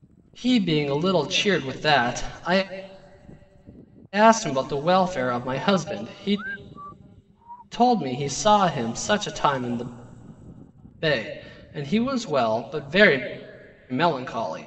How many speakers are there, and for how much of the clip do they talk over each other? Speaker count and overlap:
1, no overlap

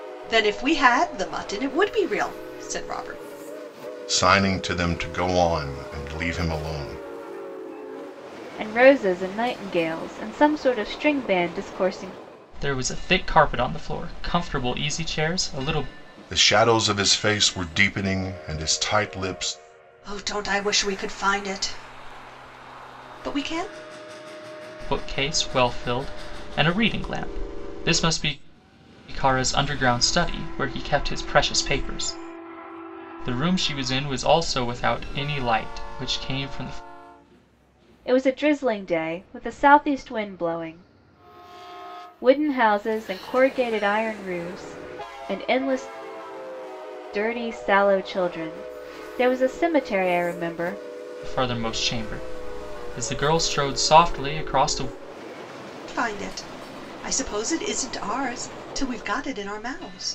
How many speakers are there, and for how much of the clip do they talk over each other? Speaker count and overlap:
4, no overlap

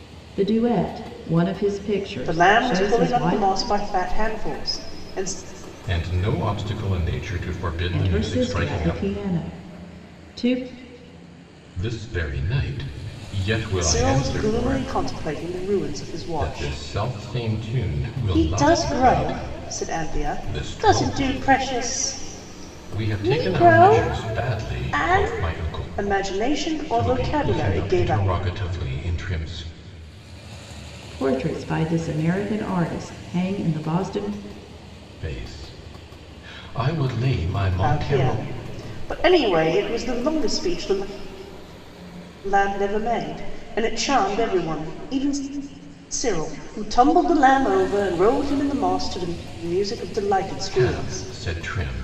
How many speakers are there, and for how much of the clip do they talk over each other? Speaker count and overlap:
3, about 21%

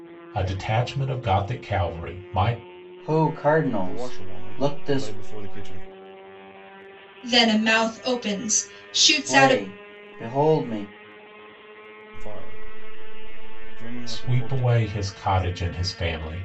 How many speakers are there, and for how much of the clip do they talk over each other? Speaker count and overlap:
4, about 15%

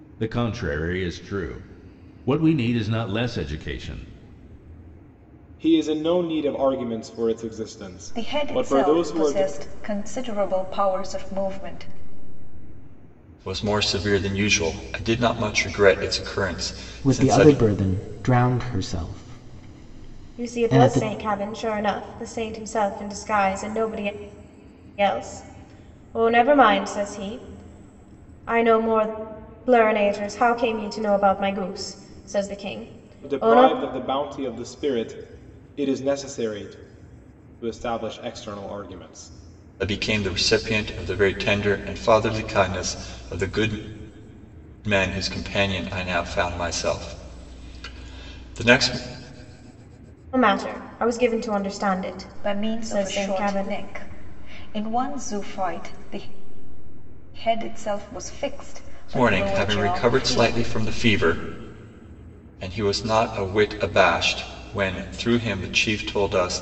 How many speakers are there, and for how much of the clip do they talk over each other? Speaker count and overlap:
6, about 9%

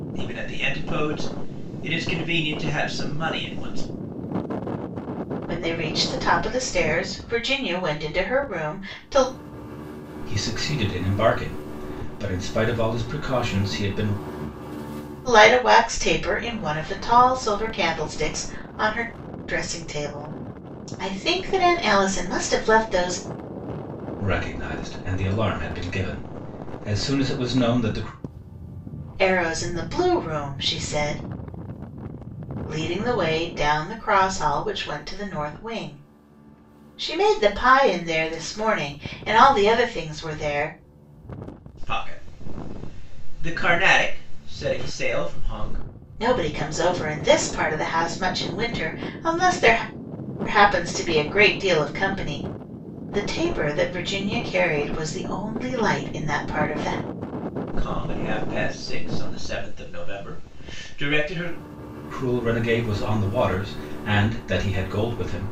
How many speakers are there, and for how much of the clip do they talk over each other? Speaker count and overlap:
3, no overlap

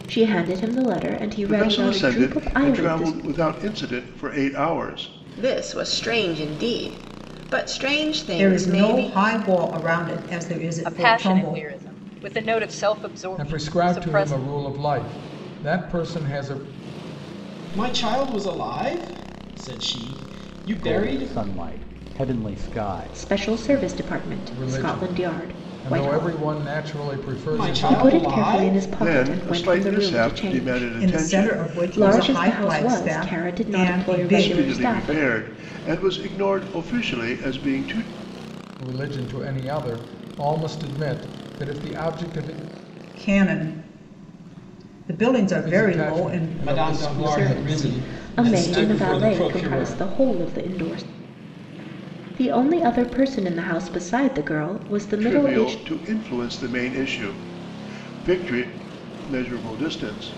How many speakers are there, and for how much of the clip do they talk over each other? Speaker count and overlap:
8, about 34%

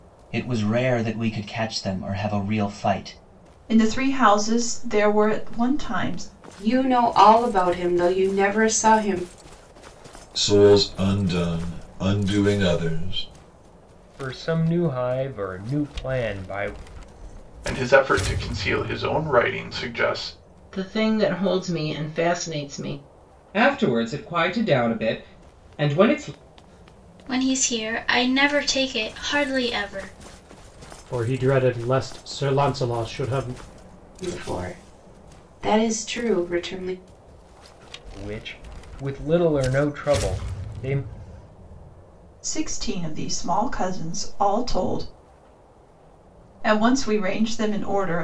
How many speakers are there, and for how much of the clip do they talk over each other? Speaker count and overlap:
10, no overlap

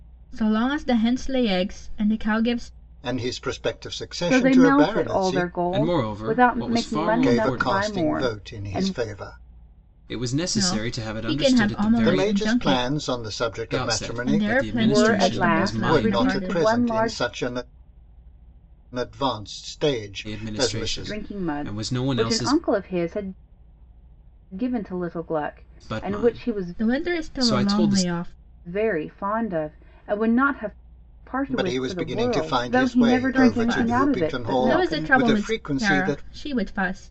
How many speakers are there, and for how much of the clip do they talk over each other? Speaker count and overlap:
4, about 53%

